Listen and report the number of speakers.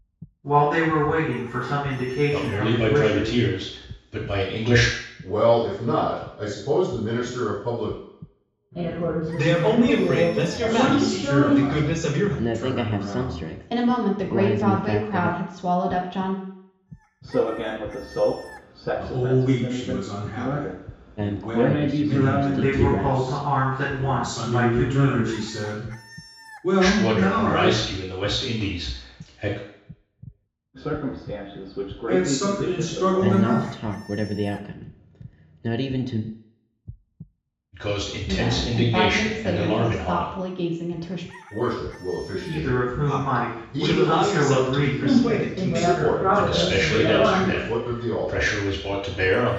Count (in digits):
9